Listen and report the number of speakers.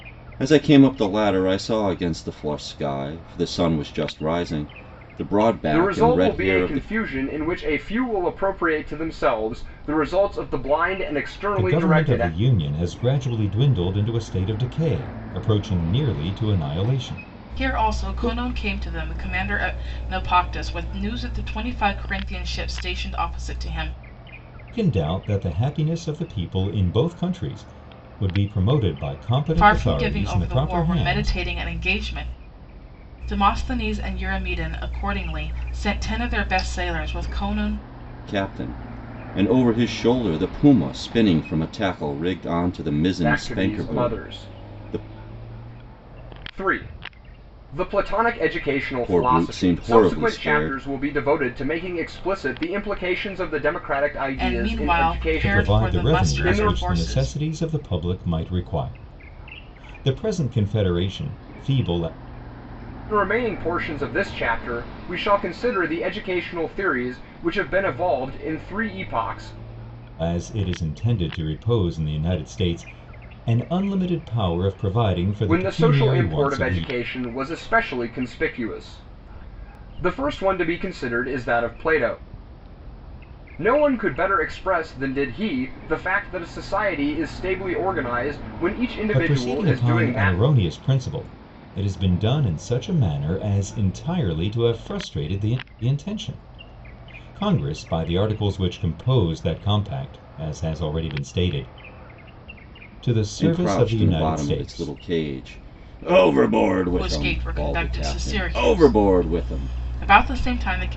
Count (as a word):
four